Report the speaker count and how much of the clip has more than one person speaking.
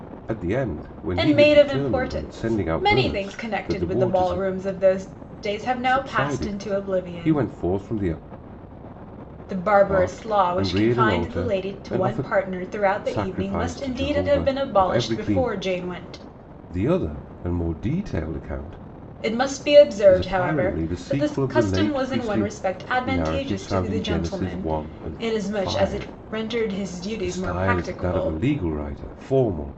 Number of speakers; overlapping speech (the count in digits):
2, about 58%